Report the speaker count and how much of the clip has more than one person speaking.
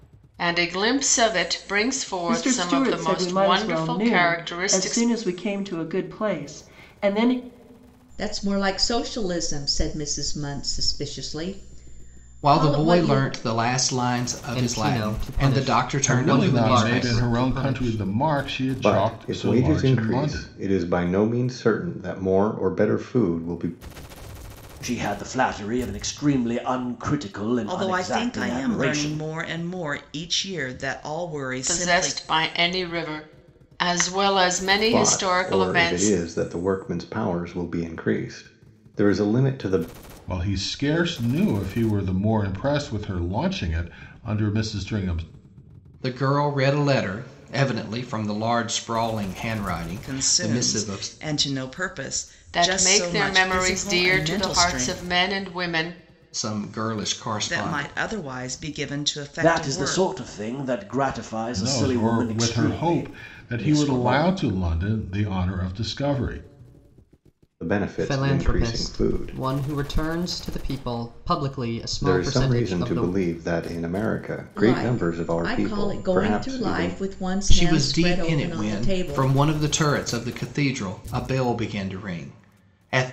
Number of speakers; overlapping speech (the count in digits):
9, about 33%